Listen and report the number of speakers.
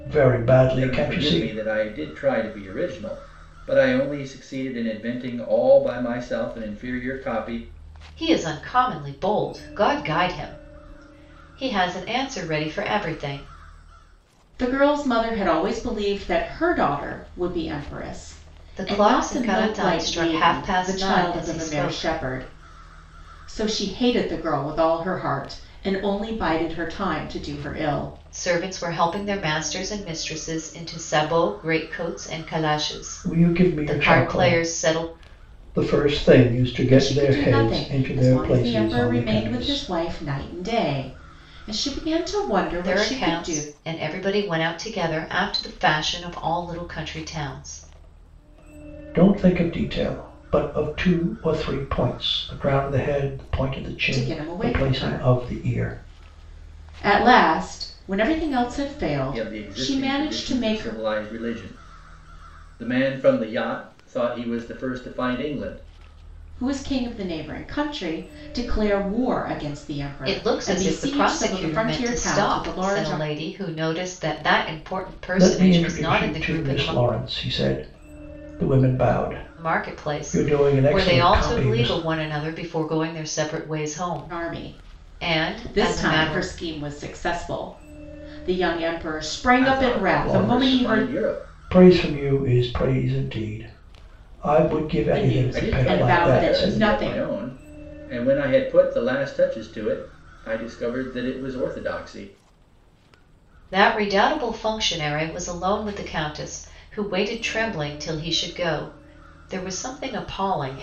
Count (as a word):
four